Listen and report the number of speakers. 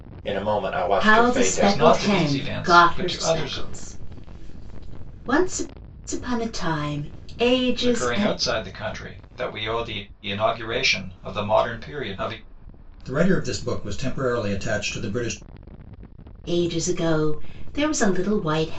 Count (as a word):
three